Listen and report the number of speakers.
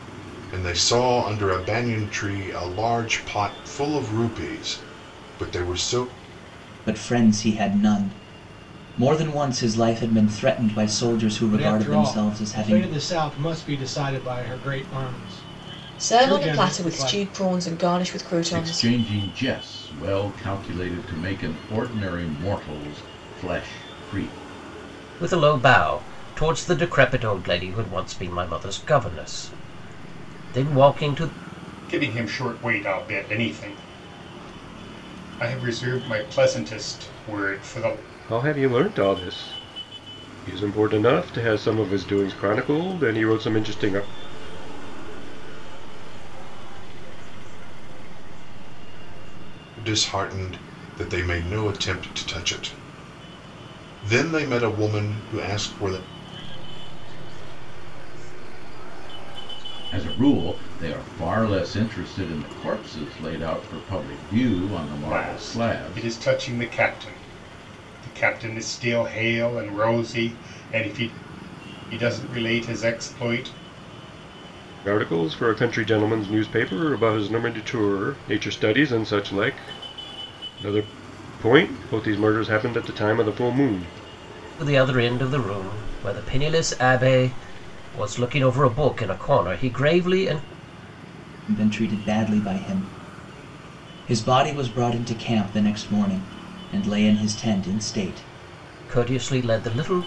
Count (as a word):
nine